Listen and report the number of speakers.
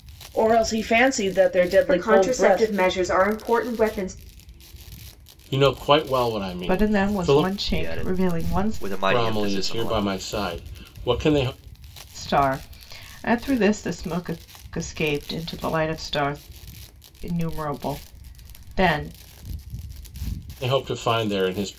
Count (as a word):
five